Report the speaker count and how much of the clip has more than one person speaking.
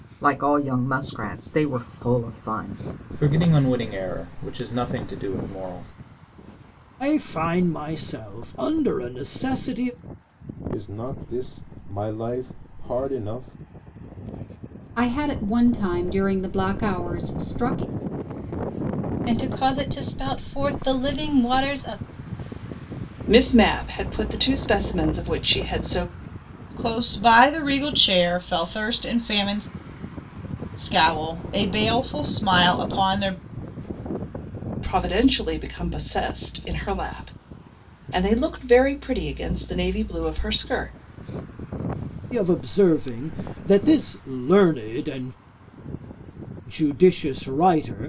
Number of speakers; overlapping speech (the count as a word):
eight, no overlap